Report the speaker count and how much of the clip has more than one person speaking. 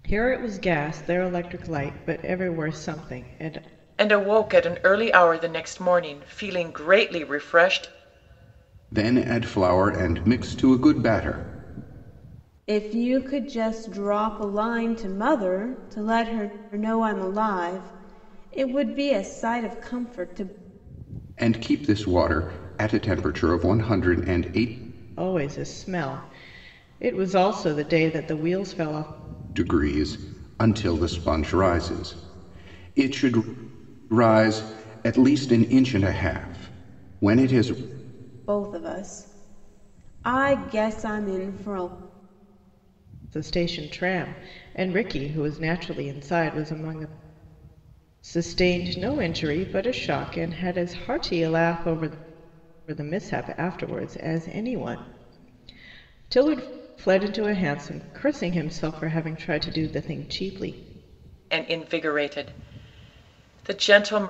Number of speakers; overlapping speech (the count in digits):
4, no overlap